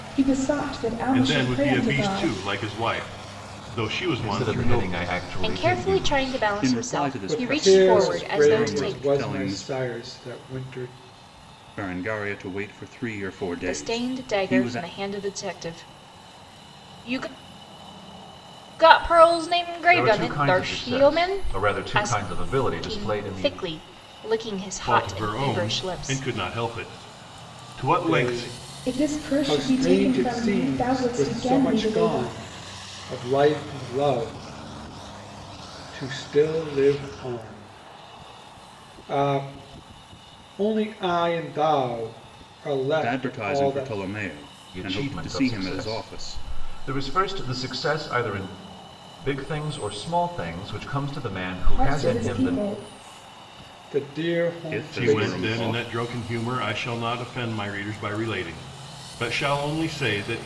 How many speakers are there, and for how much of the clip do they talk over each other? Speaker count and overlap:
six, about 35%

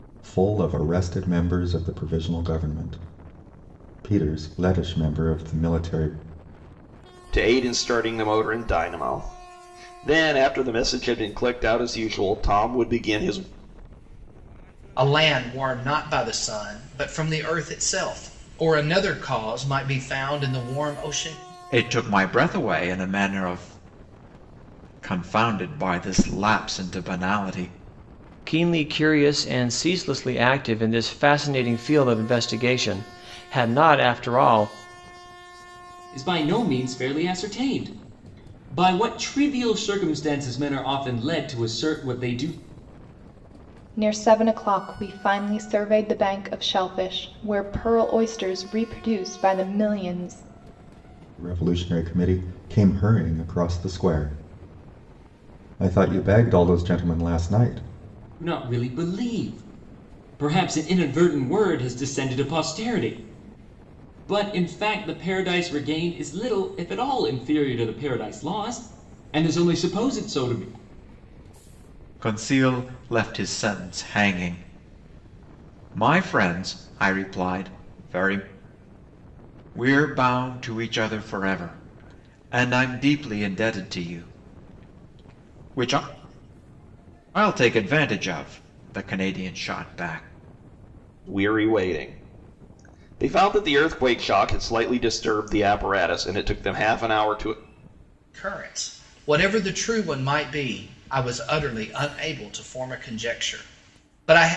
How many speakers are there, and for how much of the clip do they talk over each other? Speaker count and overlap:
seven, no overlap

